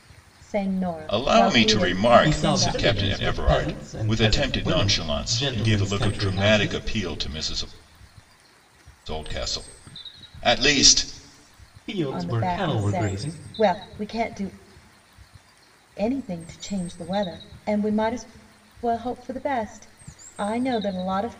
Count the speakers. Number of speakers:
3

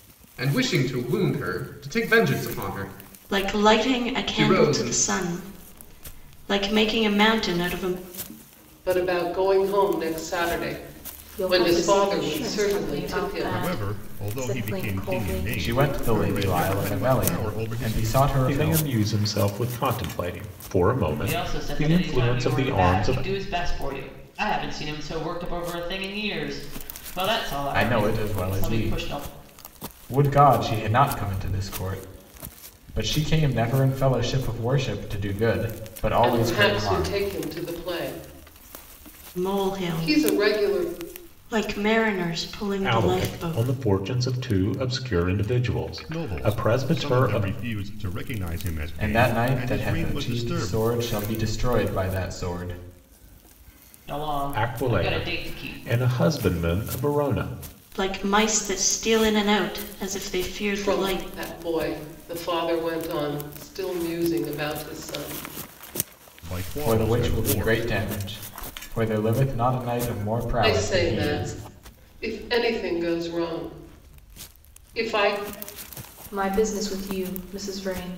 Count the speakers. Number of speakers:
8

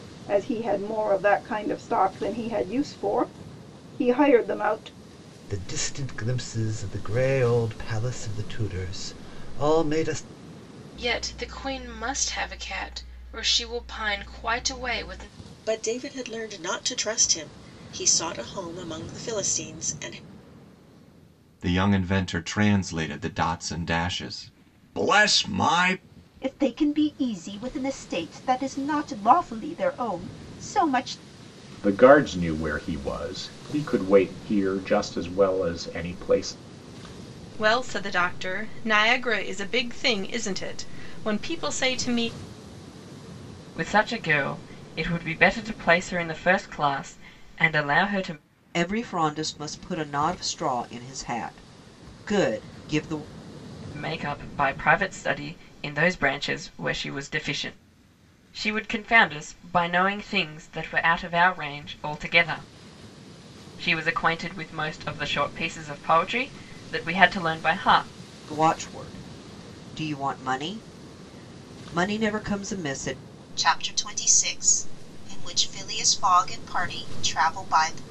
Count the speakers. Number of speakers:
10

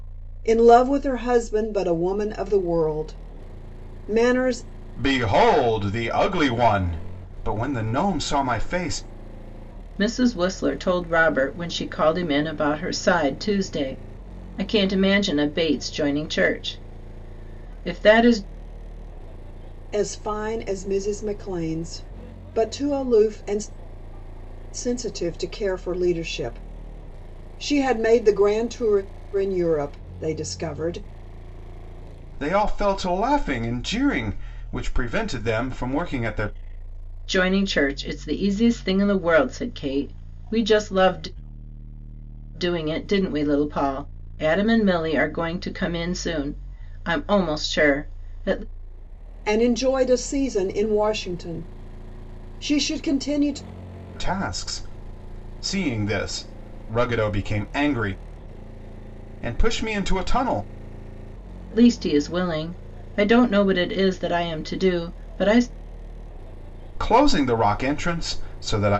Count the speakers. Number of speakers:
3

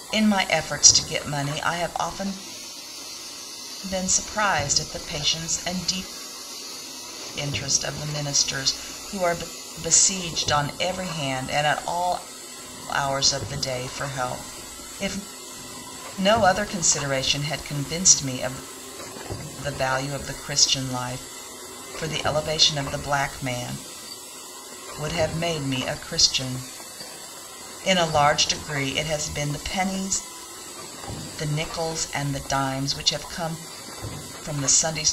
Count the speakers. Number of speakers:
1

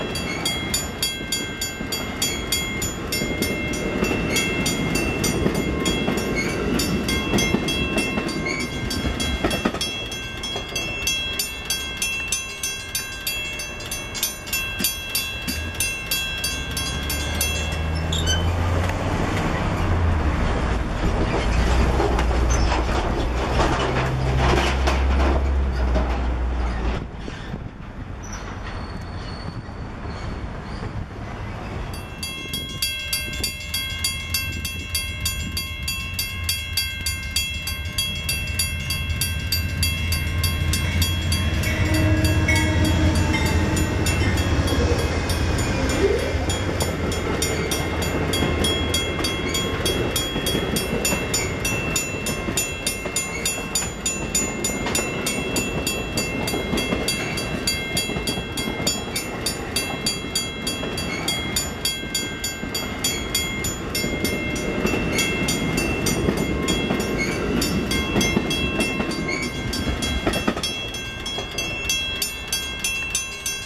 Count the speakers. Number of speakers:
0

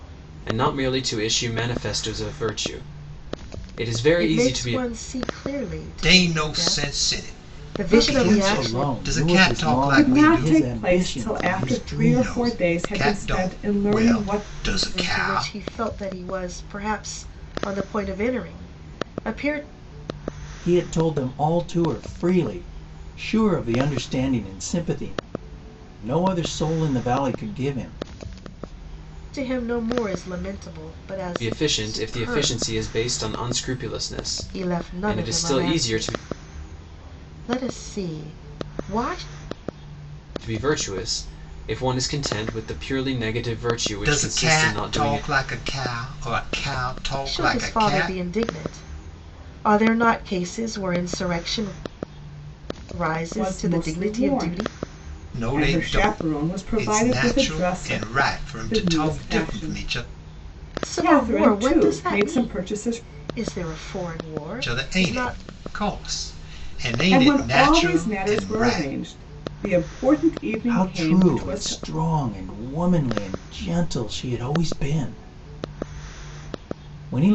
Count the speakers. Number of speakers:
5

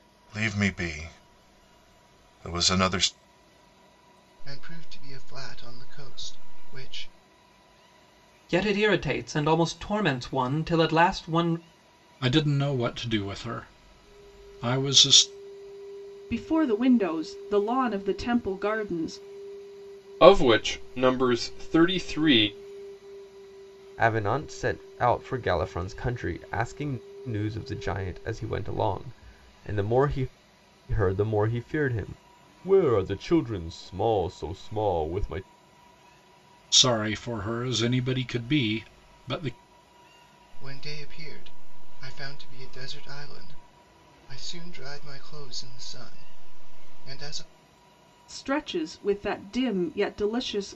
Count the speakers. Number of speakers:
7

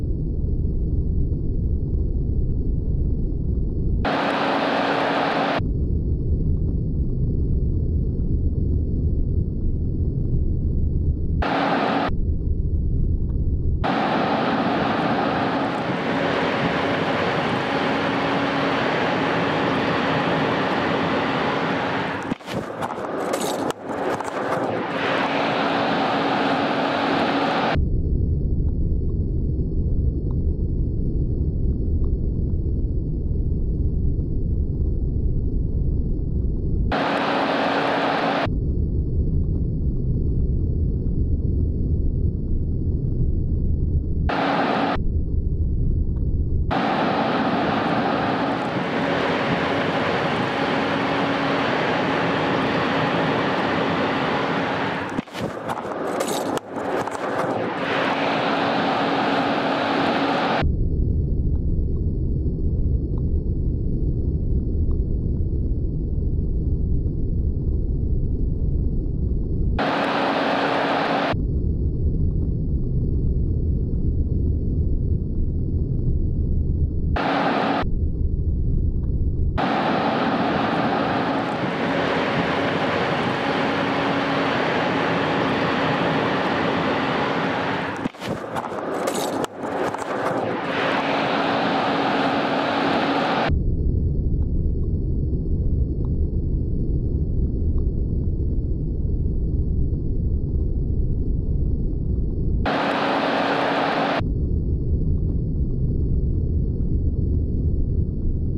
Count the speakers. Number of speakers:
0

